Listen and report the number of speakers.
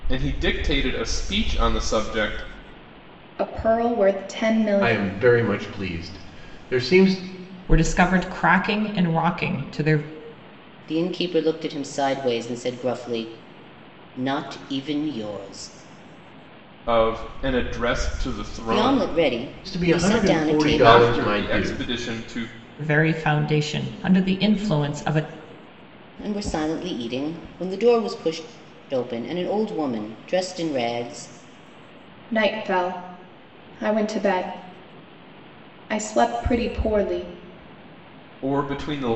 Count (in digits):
5